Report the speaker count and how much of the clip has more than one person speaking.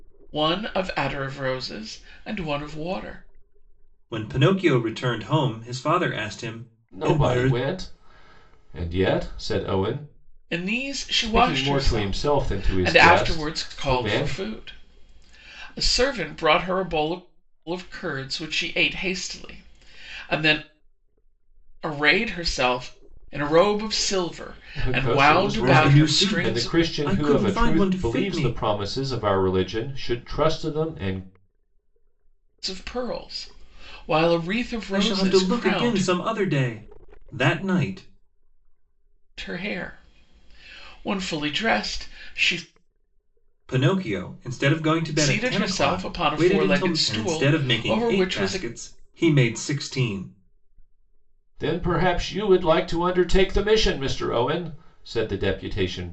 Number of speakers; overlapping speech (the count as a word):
three, about 22%